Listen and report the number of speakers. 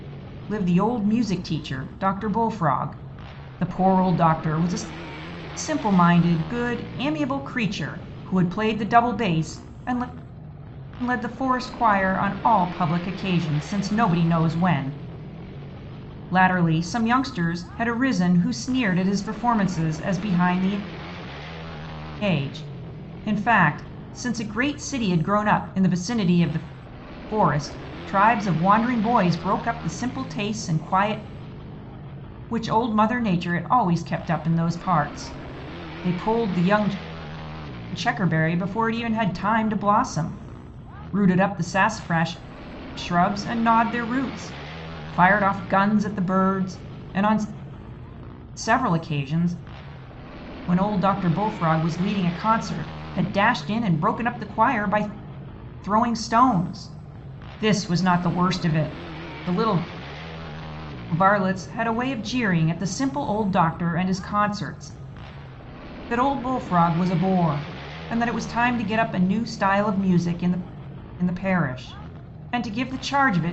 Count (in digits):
1